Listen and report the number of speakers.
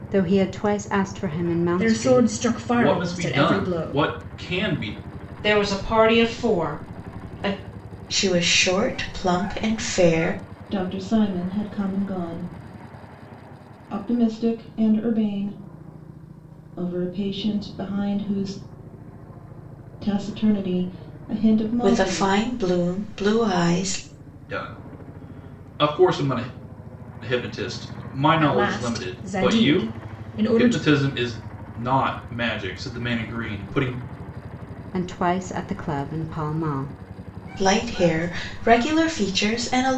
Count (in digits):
6